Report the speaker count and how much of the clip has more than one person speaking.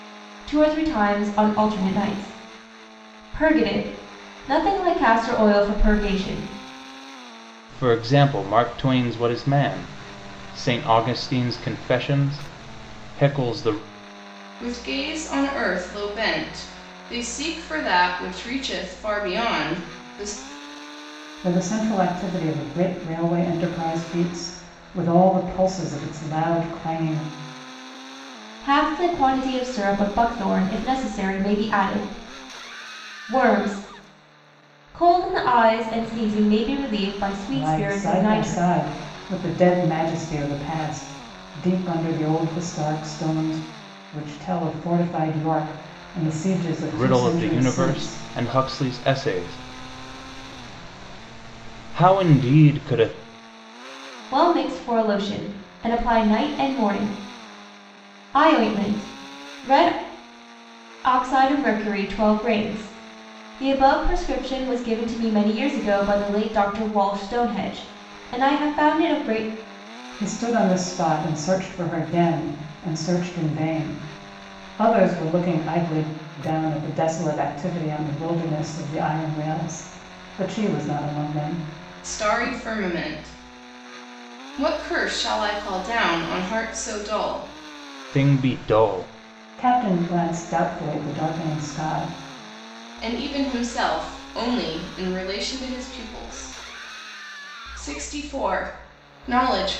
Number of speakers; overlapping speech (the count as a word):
four, about 3%